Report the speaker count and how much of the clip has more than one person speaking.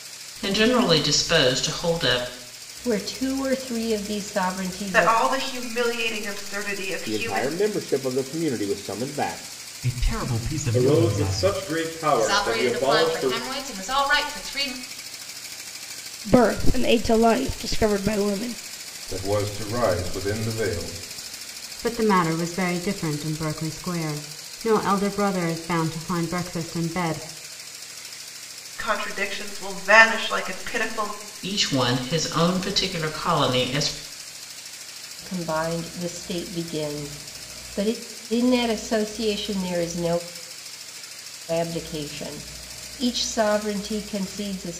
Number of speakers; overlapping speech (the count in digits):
10, about 7%